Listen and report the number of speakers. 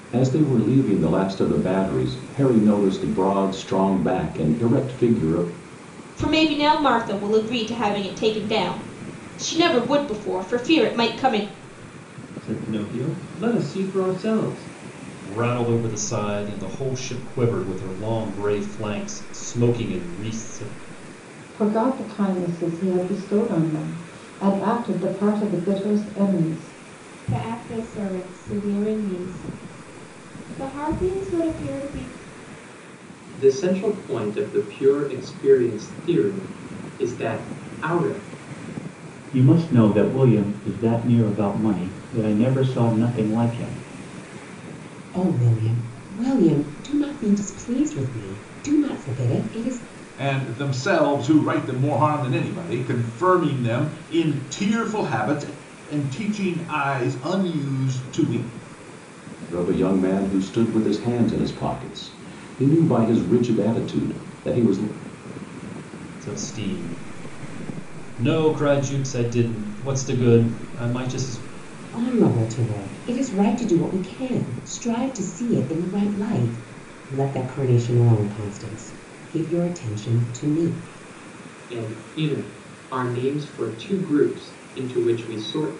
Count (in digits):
10